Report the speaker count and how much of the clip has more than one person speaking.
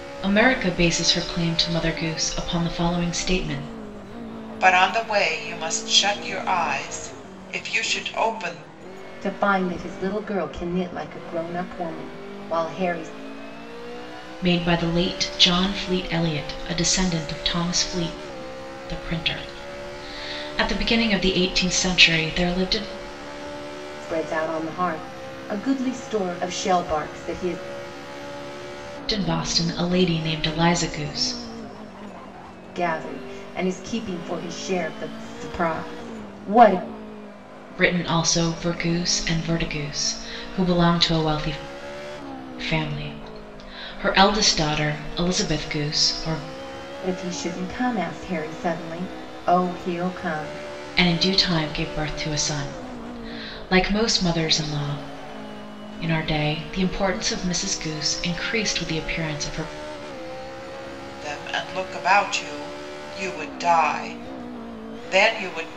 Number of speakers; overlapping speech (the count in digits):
3, no overlap